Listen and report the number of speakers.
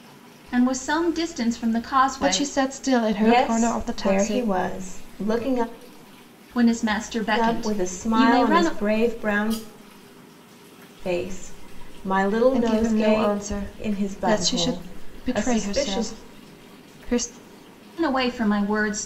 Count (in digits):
3